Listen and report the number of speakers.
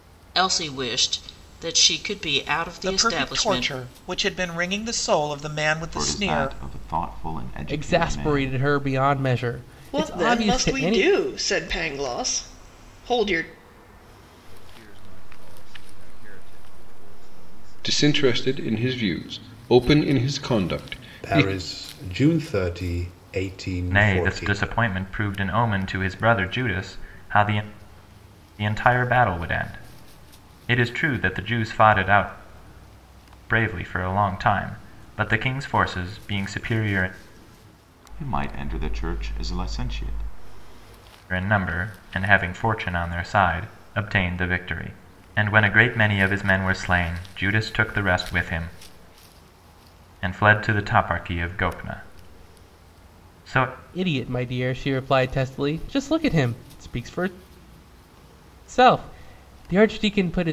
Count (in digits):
9